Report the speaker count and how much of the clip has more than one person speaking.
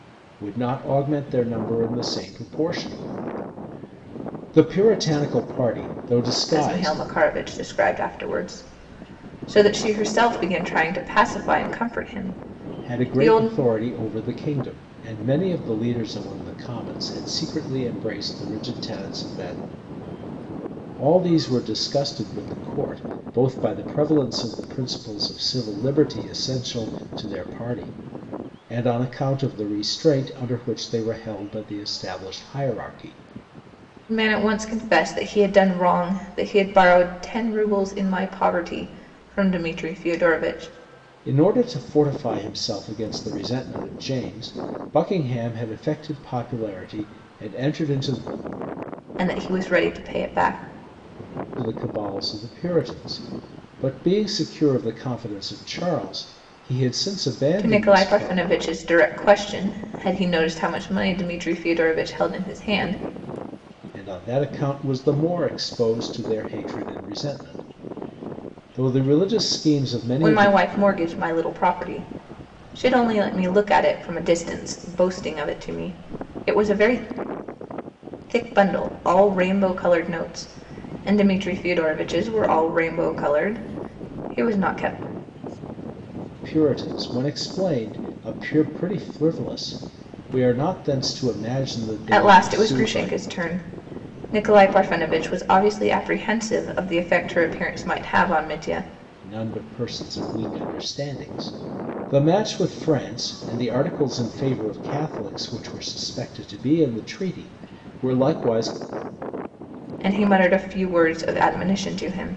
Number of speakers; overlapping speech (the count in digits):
2, about 3%